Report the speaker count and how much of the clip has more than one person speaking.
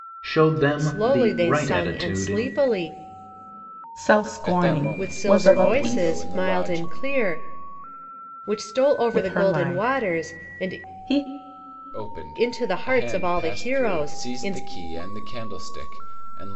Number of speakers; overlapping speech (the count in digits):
4, about 50%